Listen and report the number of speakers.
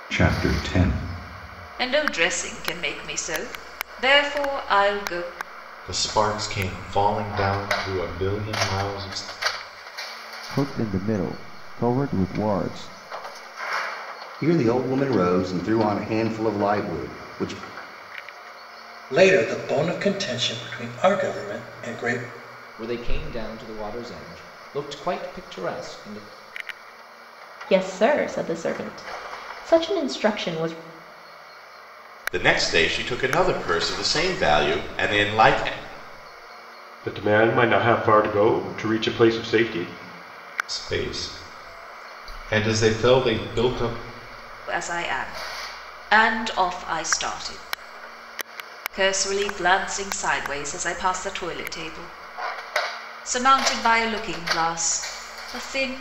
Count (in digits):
10